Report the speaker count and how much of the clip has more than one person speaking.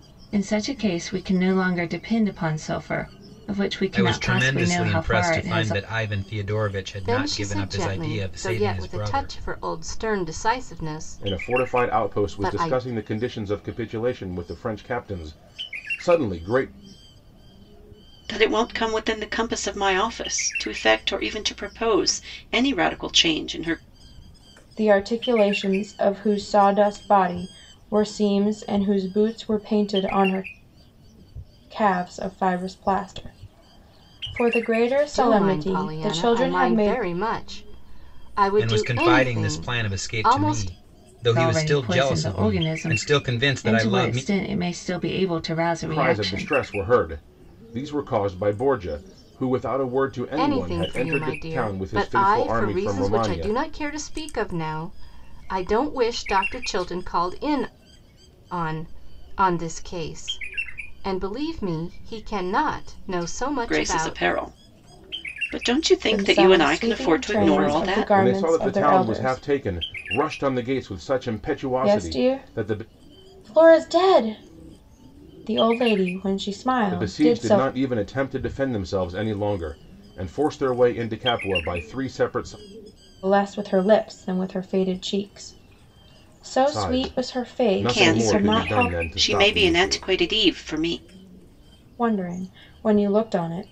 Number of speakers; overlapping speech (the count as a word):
six, about 28%